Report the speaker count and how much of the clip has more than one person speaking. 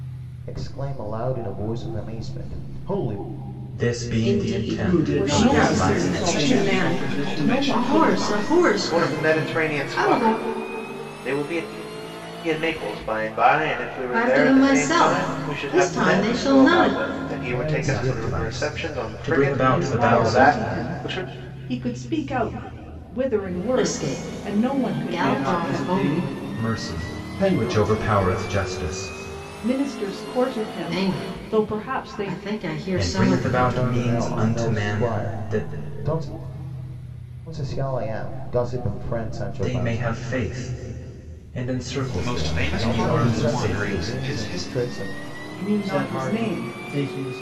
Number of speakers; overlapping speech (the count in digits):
8, about 54%